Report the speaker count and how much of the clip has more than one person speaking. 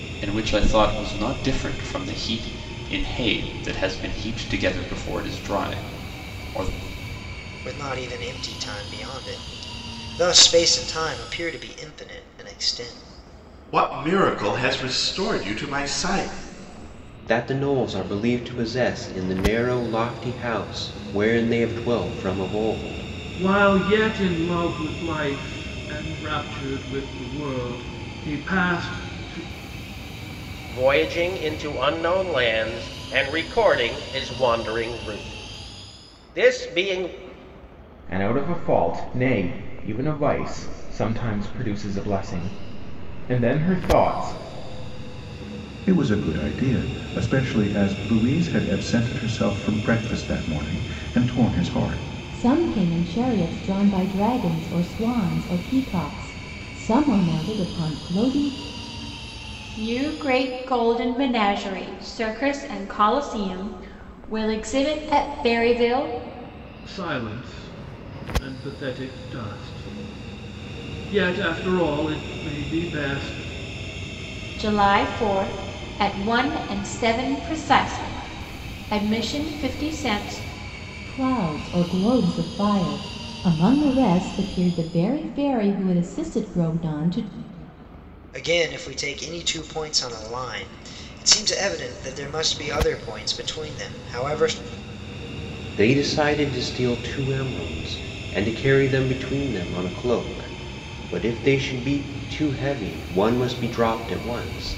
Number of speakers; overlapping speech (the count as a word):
ten, no overlap